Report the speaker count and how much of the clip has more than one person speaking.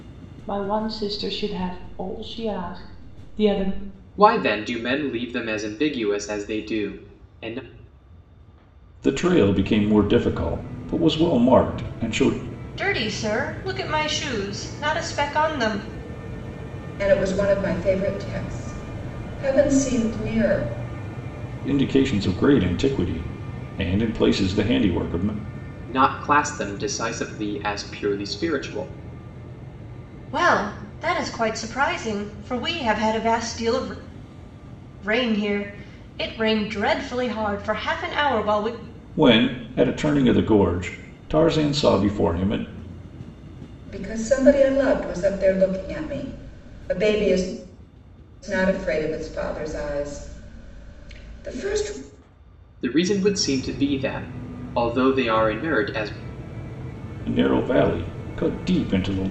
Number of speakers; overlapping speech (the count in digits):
5, no overlap